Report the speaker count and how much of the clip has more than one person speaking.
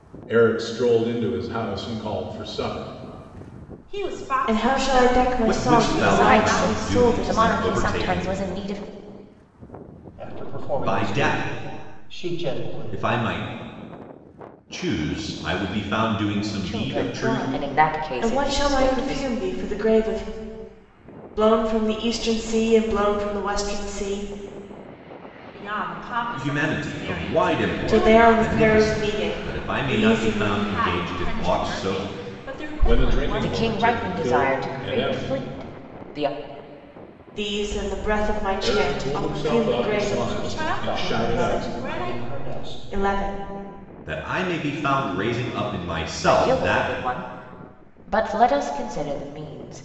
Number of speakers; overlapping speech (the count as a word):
six, about 44%